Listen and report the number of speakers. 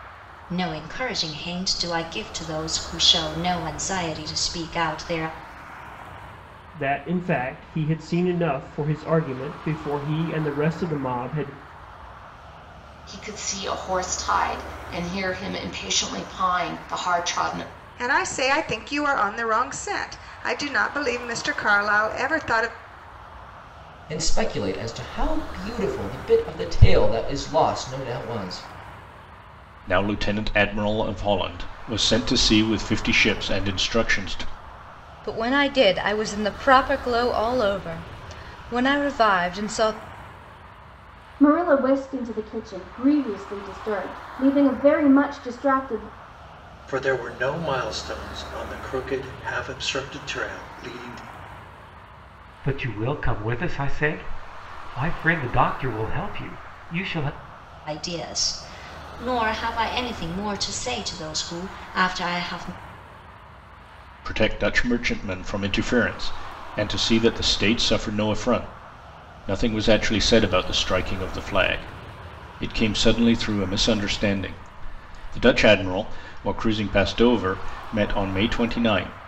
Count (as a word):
ten